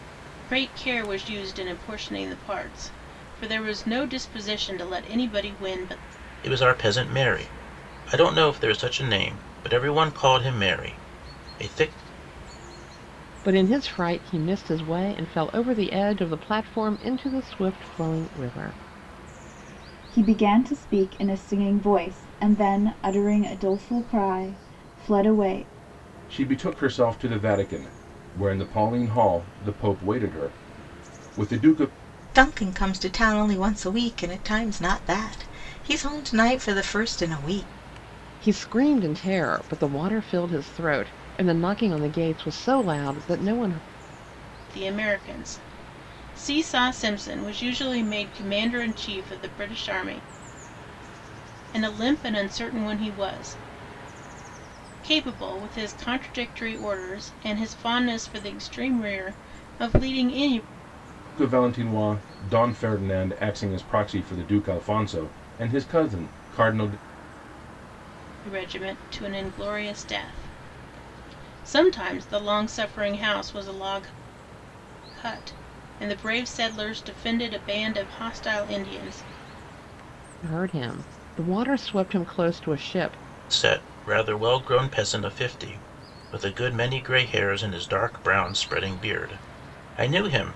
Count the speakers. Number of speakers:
6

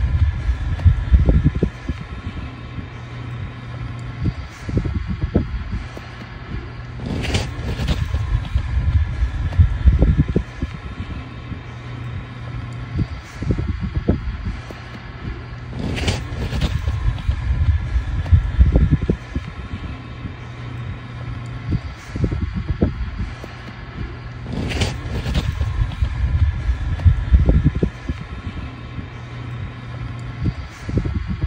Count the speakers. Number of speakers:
0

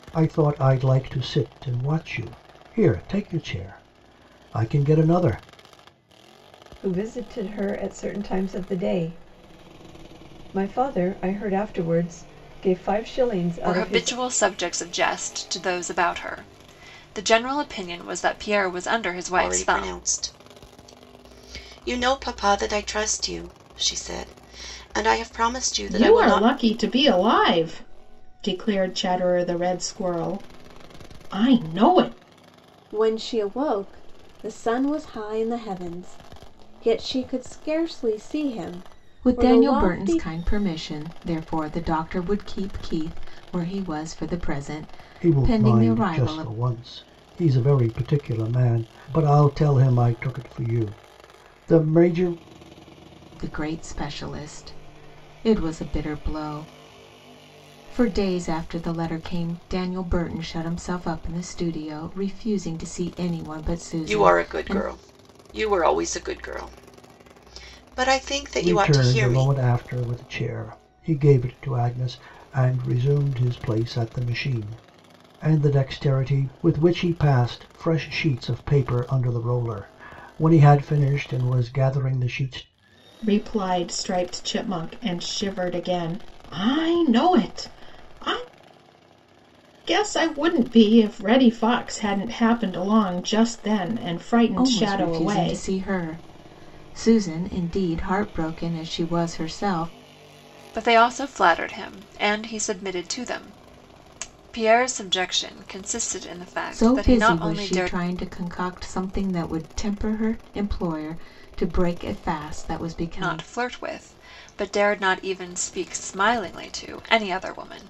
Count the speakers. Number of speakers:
7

